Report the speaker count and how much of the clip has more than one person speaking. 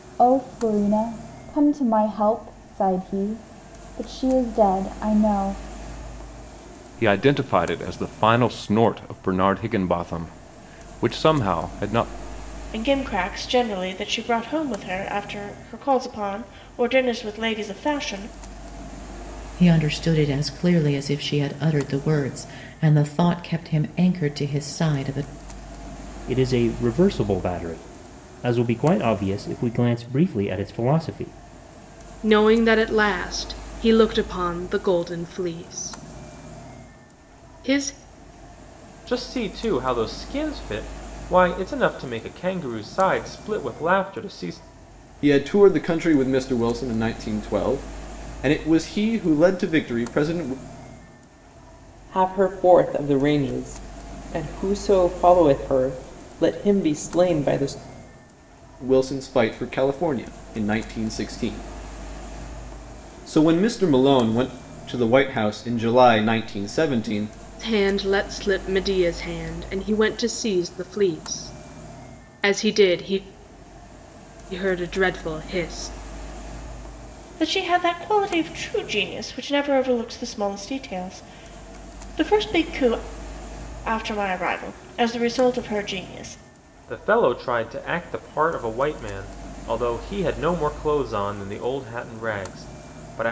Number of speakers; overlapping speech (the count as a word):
nine, no overlap